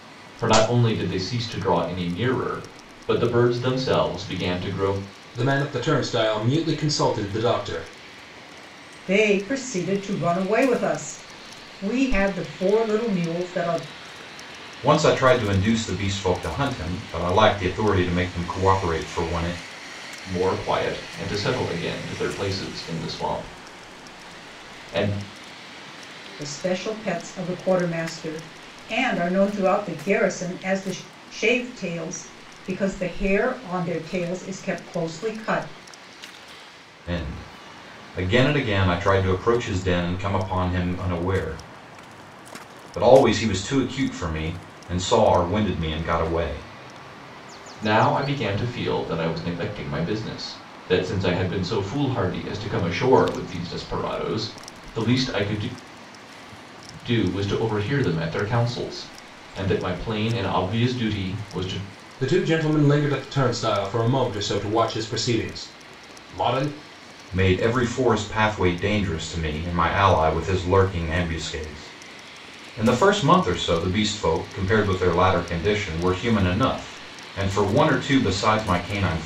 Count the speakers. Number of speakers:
four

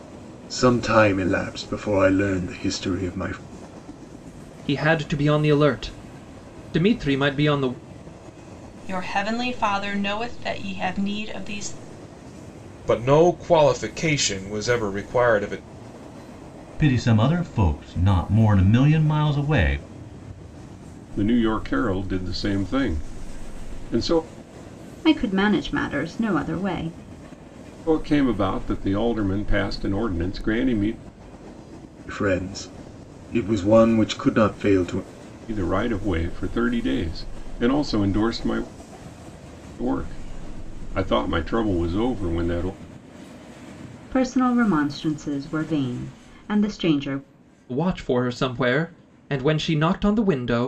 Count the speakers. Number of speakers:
seven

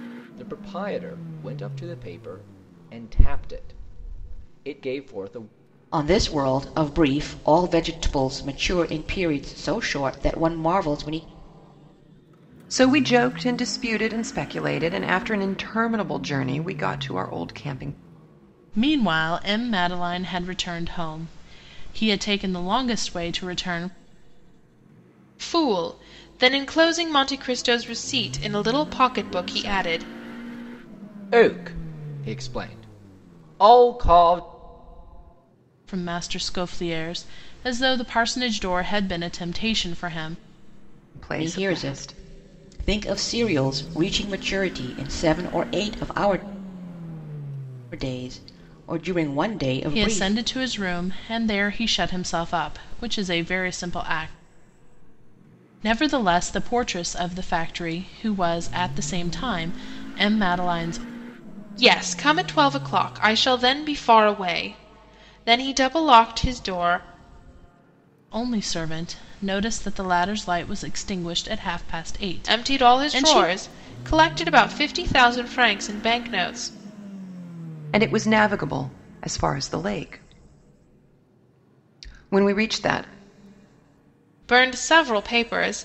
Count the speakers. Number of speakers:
five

